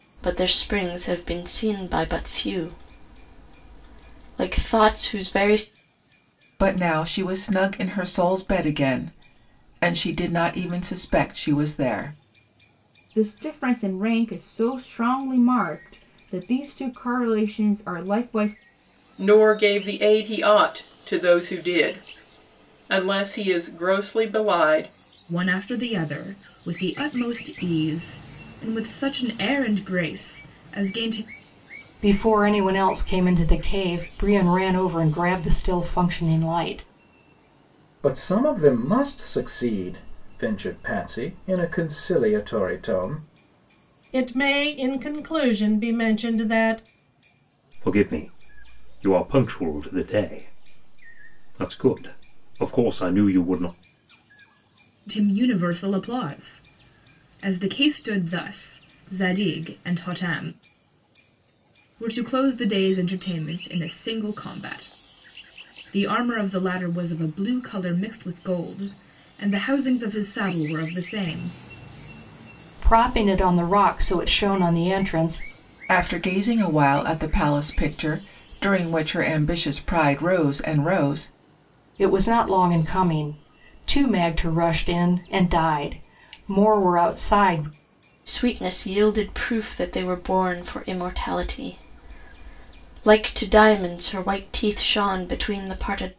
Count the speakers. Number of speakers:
9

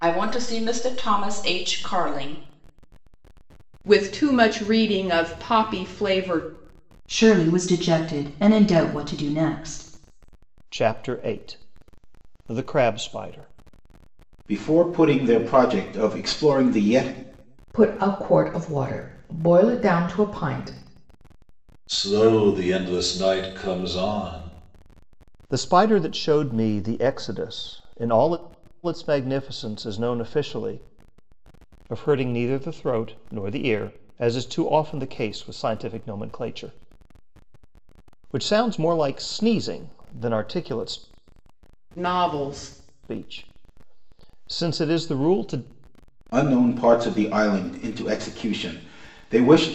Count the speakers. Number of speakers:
7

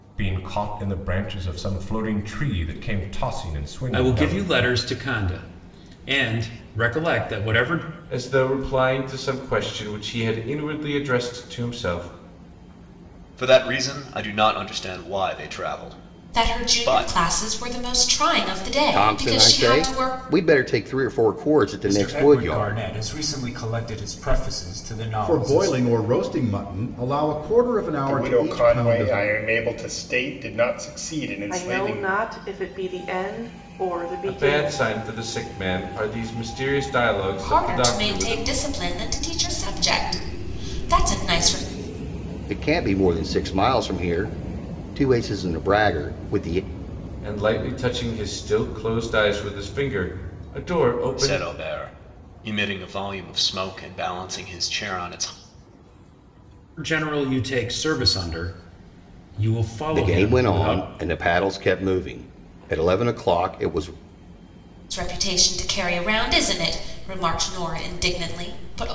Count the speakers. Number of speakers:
10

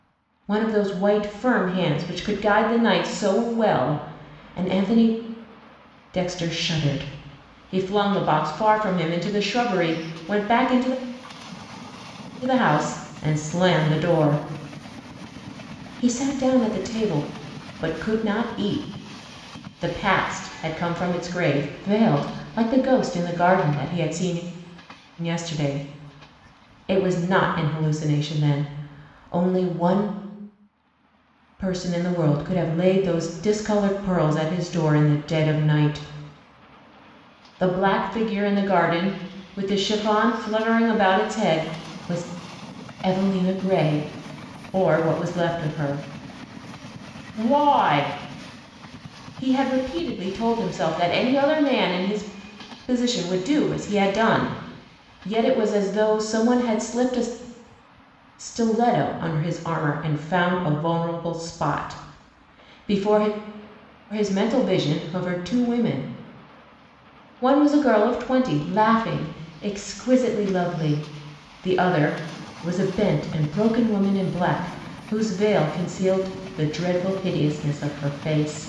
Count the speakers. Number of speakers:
1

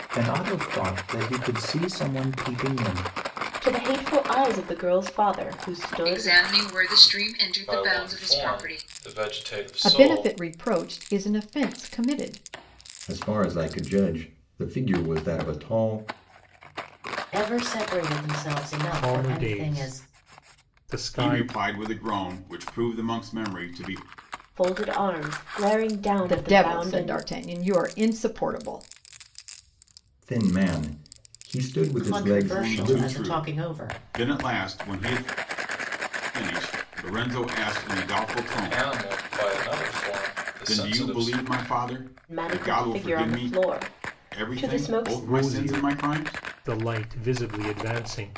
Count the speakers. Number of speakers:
9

